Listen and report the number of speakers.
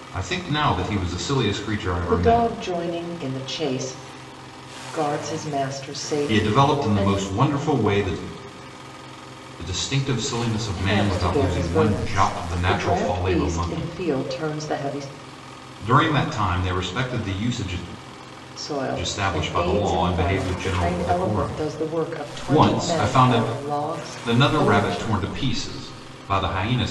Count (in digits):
2